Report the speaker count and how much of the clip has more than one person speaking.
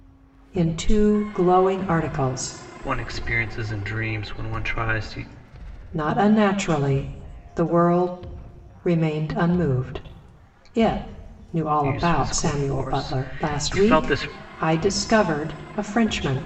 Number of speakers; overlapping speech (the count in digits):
2, about 15%